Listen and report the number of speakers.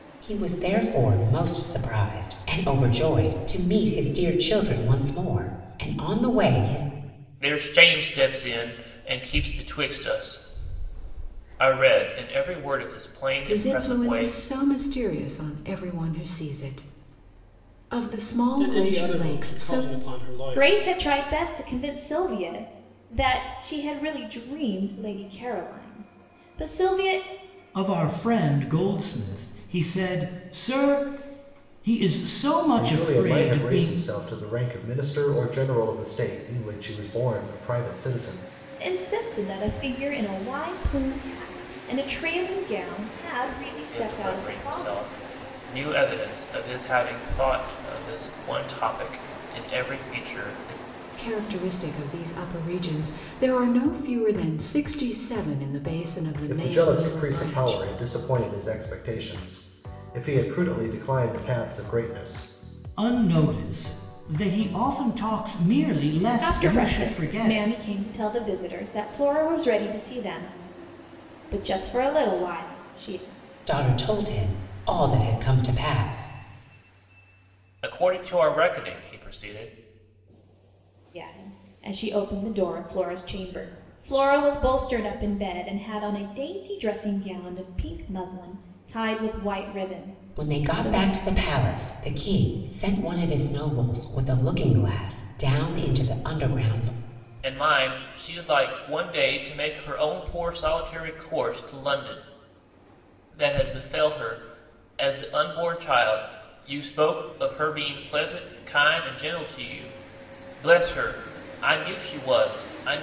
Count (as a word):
seven